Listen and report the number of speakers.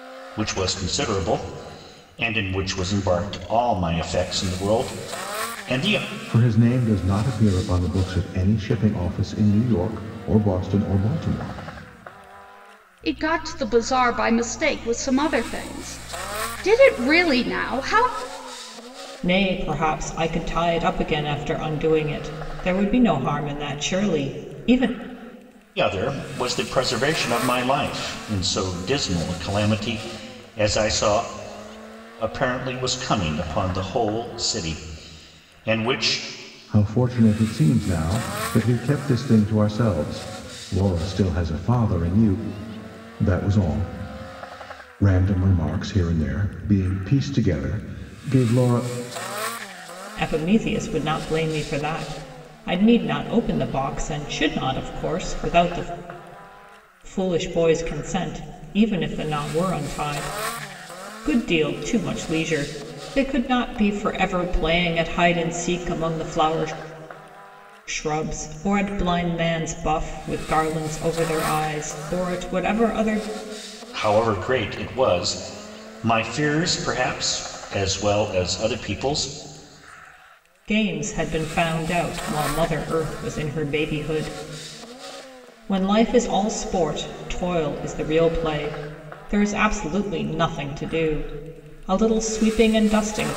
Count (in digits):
4